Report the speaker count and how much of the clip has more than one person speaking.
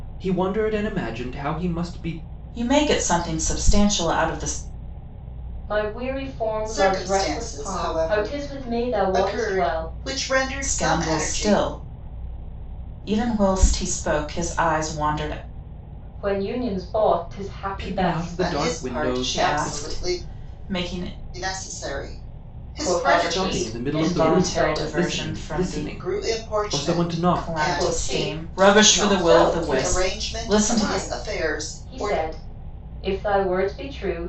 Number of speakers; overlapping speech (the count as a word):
four, about 45%